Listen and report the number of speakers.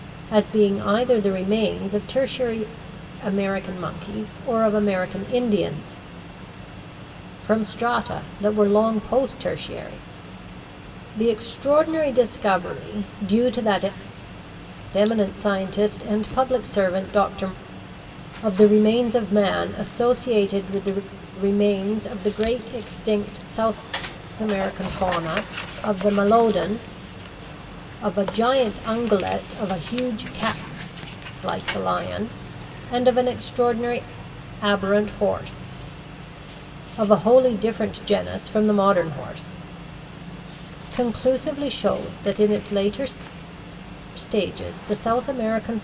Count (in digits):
1